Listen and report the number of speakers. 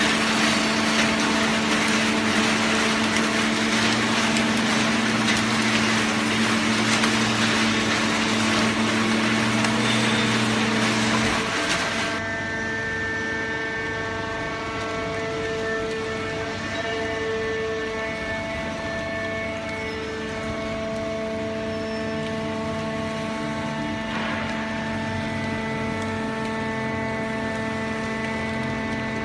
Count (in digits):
0